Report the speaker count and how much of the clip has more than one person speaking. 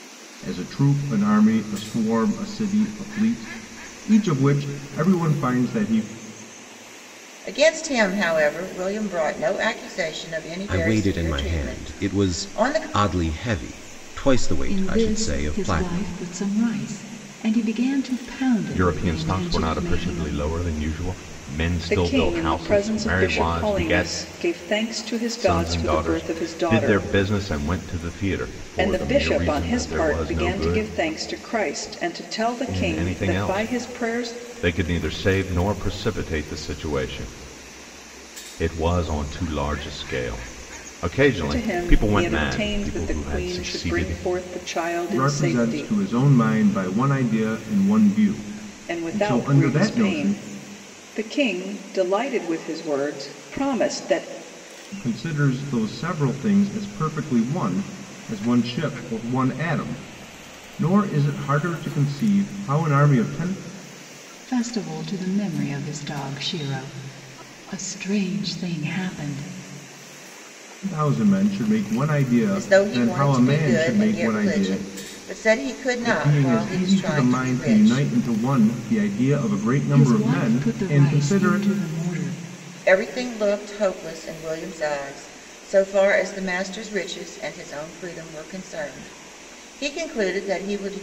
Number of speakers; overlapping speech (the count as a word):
six, about 27%